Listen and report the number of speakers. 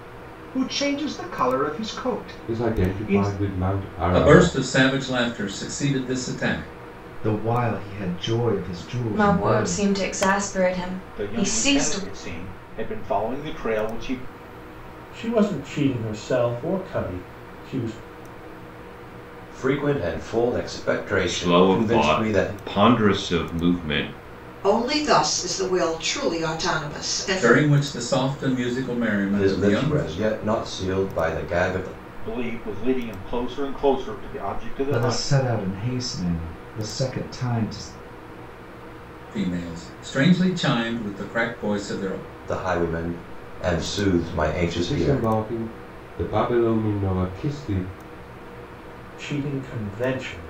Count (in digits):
10